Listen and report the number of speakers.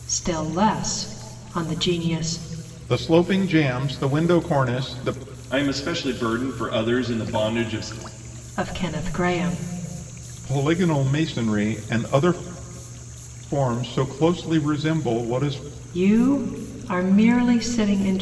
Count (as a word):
three